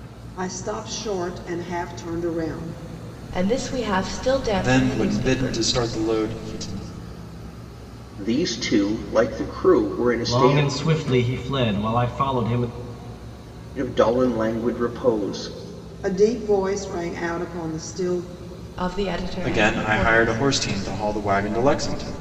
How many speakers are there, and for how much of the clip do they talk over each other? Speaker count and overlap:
5, about 11%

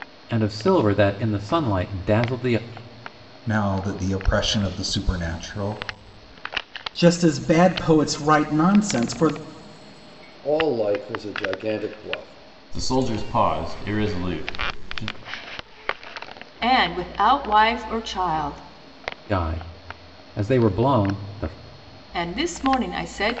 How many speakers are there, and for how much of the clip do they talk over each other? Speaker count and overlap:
6, no overlap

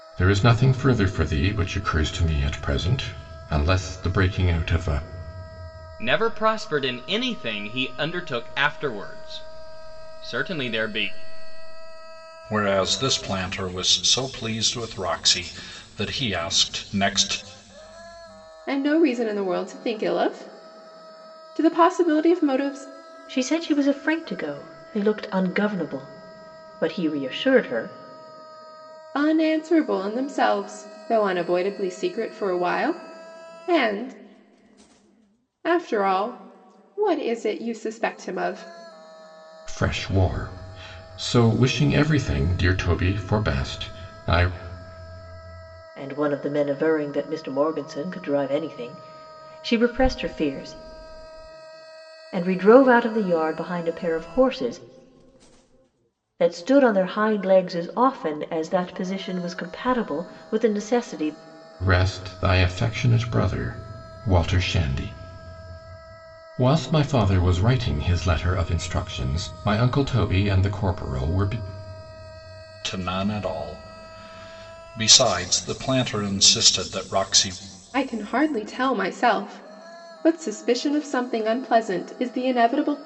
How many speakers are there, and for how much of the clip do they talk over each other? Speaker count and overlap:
5, no overlap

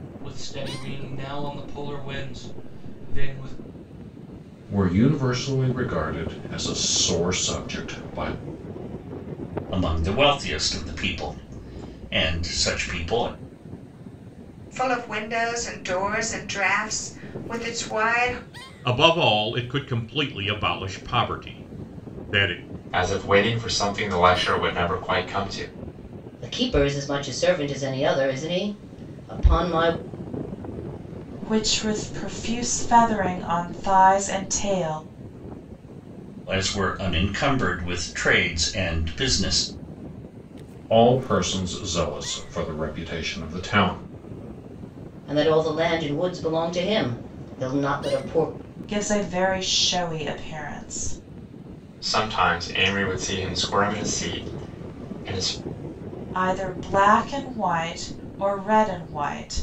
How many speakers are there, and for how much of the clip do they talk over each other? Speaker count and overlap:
8, no overlap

